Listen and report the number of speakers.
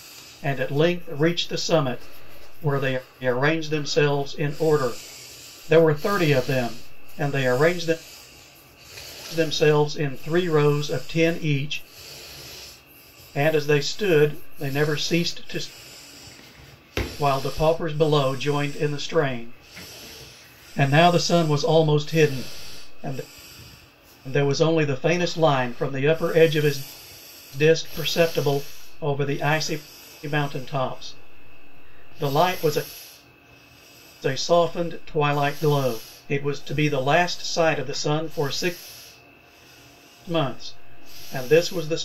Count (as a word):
one